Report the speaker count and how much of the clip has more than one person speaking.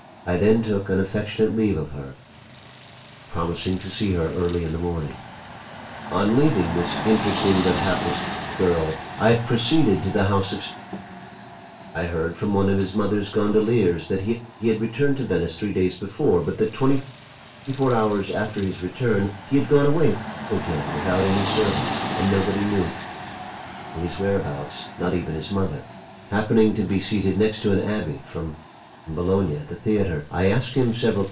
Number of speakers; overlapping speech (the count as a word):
one, no overlap